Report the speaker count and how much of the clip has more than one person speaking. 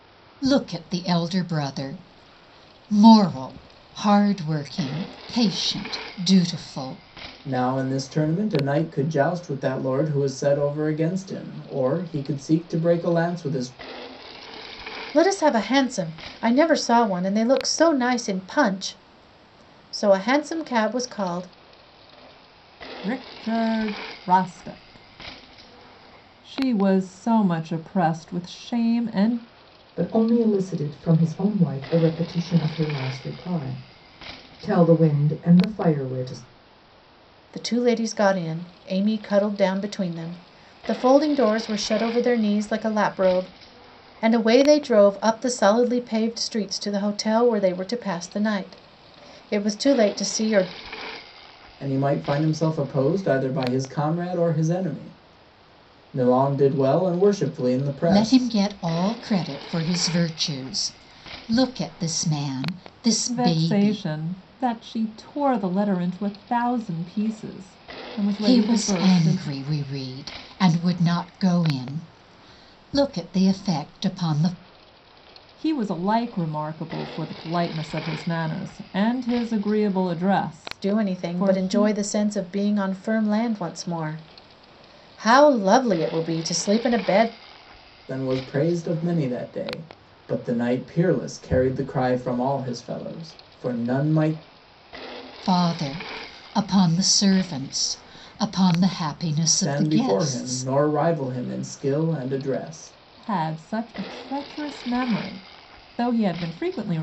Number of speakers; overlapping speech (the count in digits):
5, about 4%